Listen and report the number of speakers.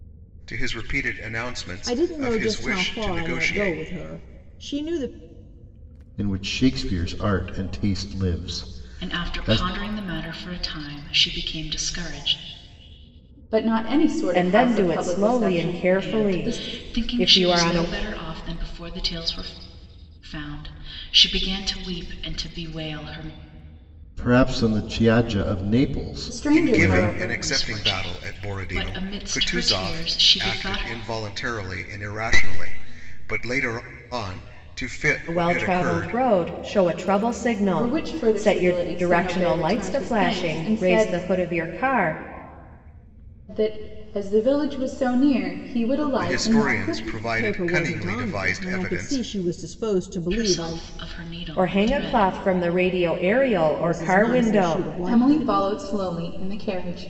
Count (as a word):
six